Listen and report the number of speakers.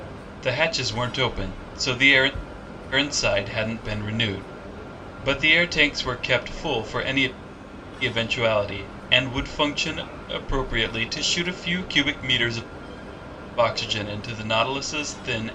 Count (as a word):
one